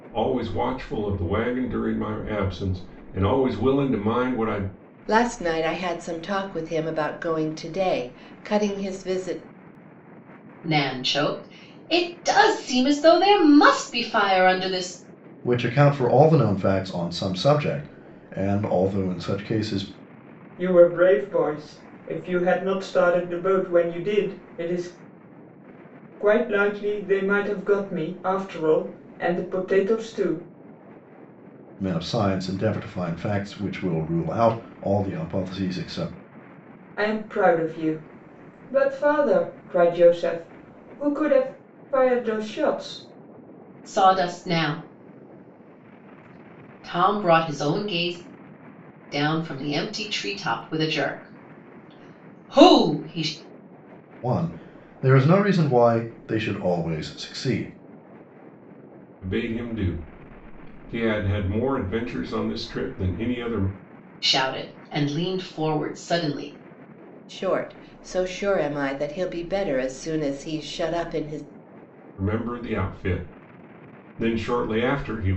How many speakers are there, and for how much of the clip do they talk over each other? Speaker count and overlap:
5, no overlap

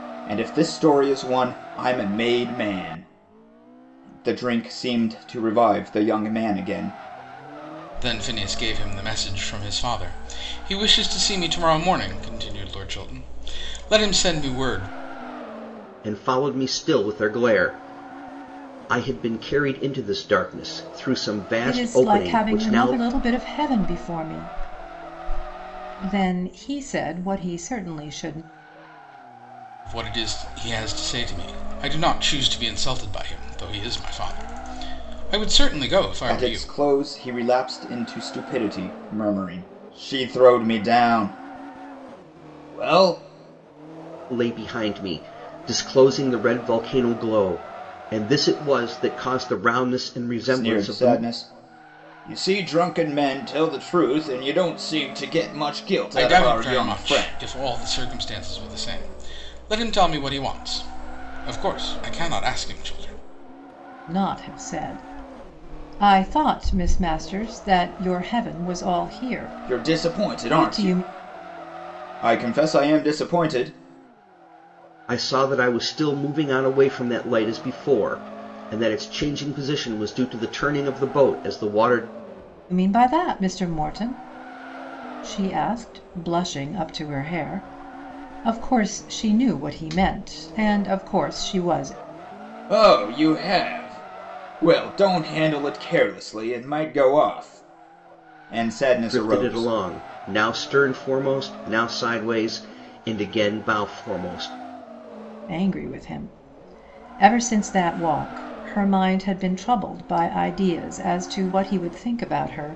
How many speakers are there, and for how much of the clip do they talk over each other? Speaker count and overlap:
4, about 5%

